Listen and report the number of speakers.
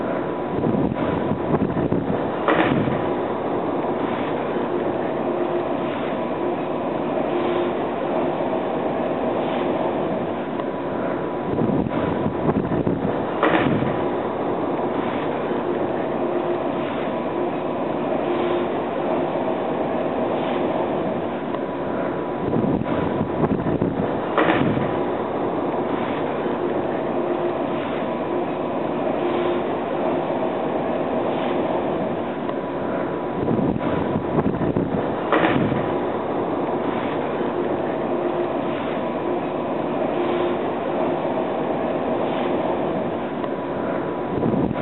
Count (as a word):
zero